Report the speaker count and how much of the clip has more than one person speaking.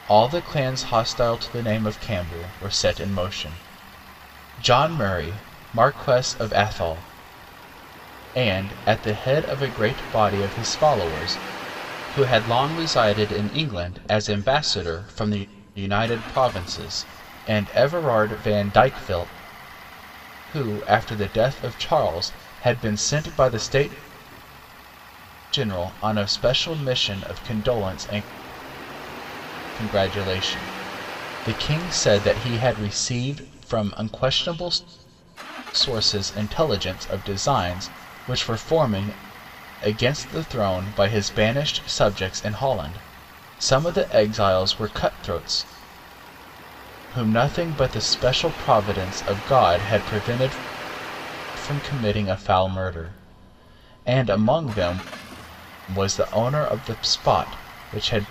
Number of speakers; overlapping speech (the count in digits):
1, no overlap